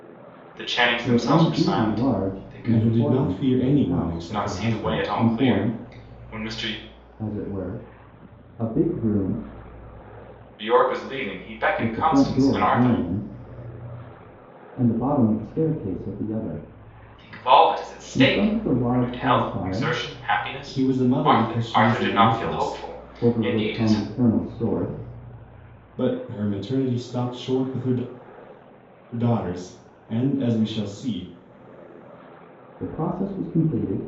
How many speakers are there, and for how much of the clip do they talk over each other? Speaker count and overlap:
three, about 32%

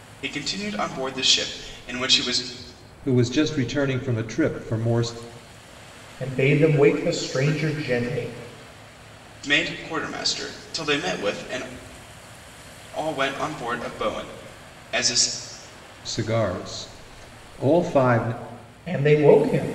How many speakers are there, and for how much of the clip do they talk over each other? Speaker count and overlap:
three, no overlap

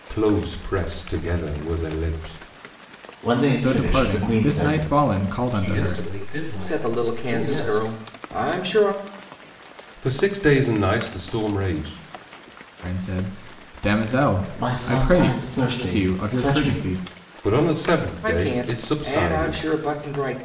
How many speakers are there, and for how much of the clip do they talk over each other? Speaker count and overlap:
five, about 30%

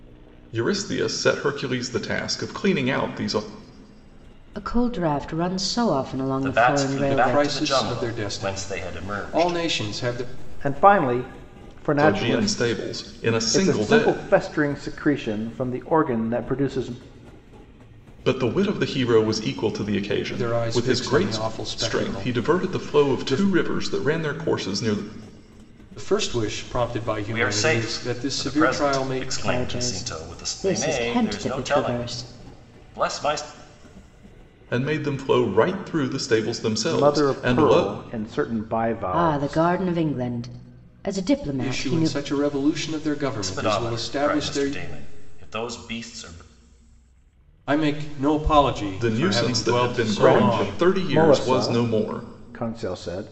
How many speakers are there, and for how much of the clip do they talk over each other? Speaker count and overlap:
five, about 38%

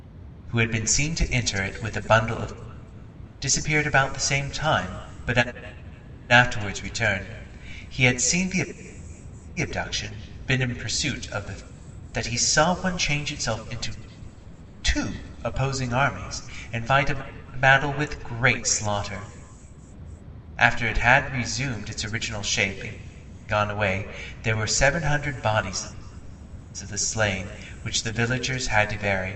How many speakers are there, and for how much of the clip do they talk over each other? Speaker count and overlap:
one, no overlap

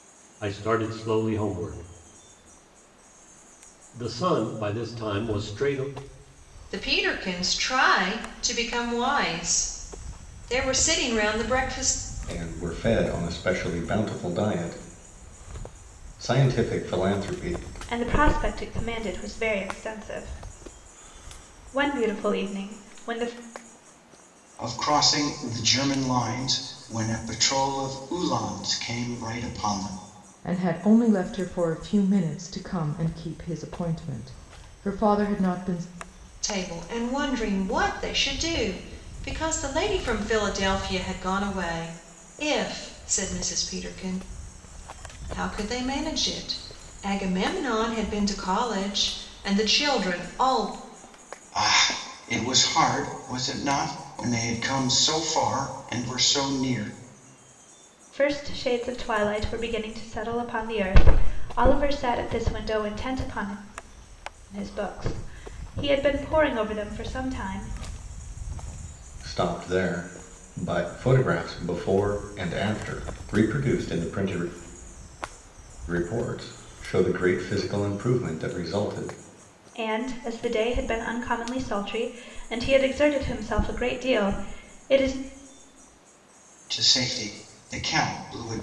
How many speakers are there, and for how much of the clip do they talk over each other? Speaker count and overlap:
six, no overlap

